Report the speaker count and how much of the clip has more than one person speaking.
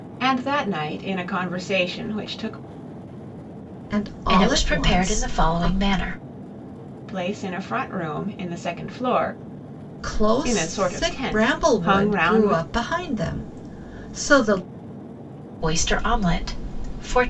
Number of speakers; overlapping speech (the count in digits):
3, about 22%